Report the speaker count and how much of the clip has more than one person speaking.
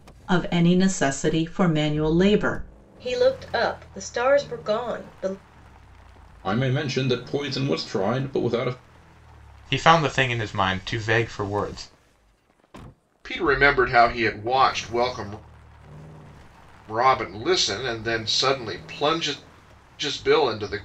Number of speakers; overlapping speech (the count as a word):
five, no overlap